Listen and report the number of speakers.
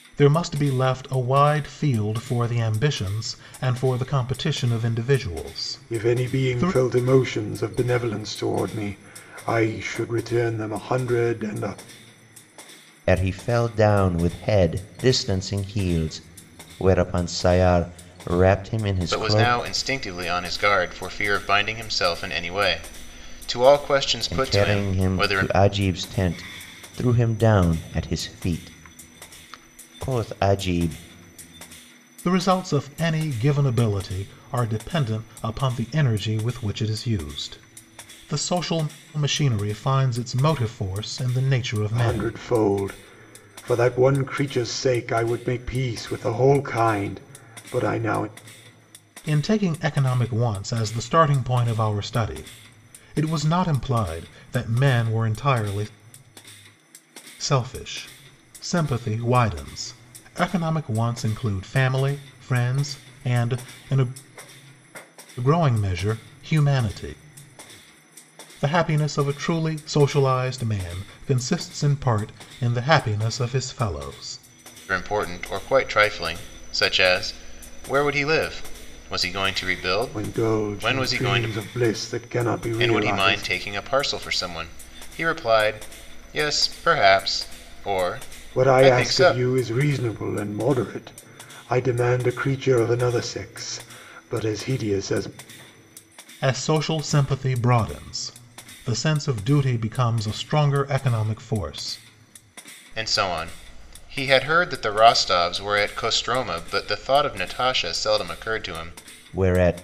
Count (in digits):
4